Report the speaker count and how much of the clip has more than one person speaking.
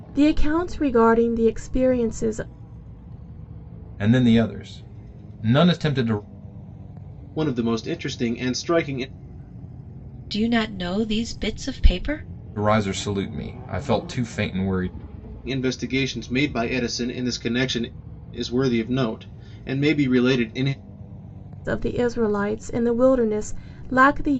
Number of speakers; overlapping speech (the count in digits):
4, no overlap